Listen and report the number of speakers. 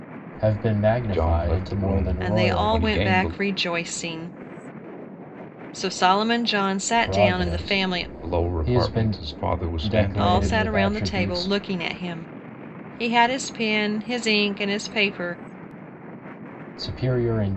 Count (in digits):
3